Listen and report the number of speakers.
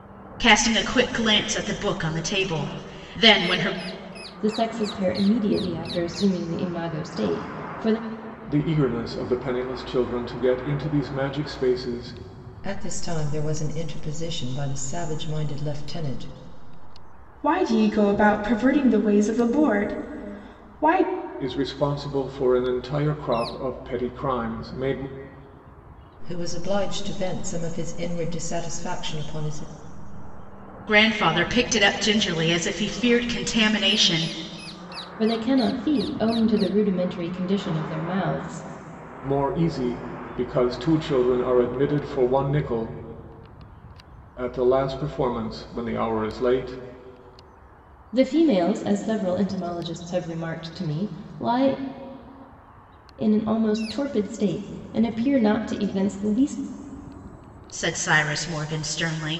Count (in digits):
5